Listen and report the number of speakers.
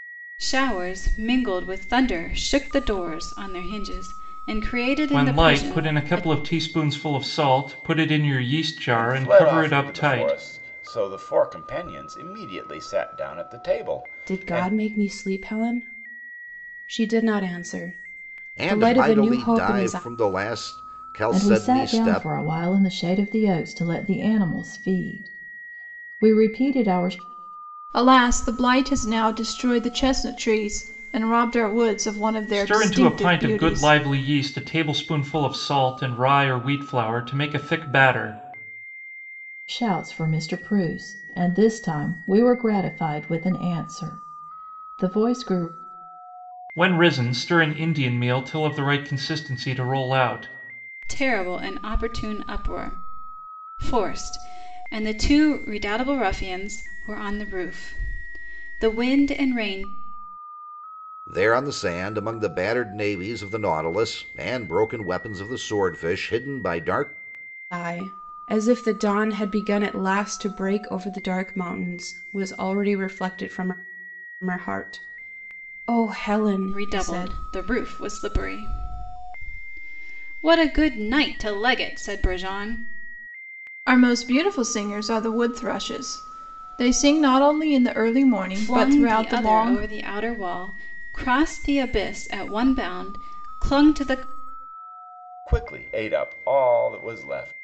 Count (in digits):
7